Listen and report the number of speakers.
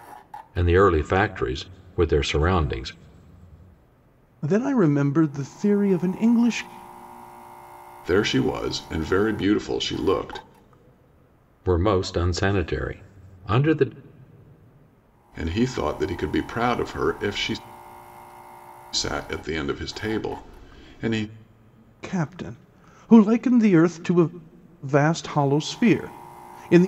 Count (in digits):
3